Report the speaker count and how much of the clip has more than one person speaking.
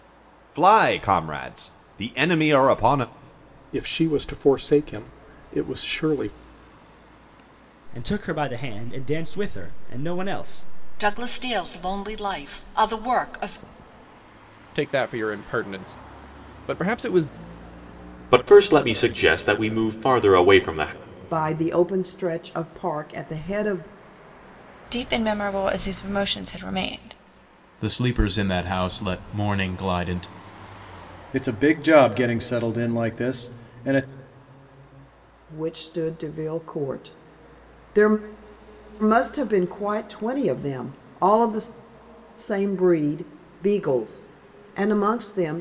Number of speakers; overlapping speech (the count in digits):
10, no overlap